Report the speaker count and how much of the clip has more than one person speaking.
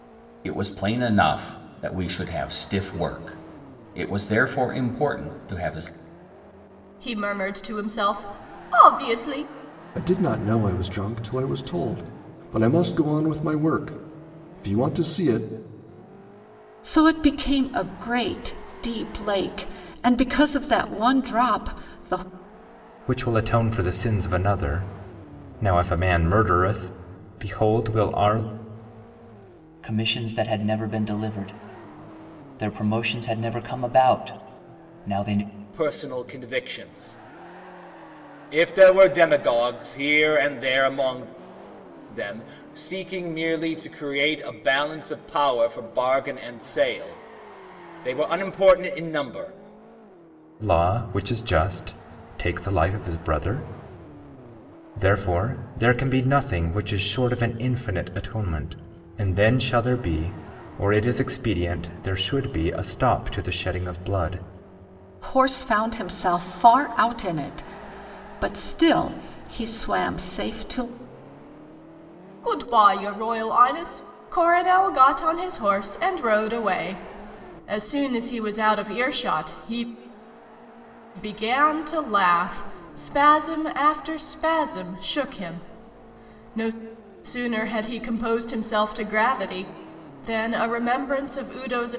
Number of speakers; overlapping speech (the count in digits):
7, no overlap